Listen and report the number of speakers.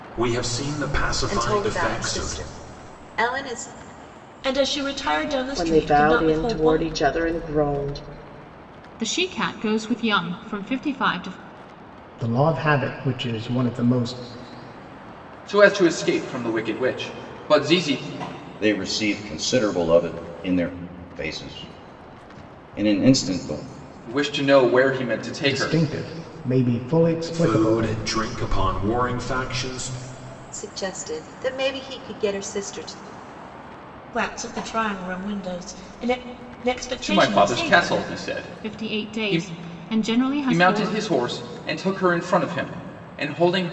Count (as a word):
eight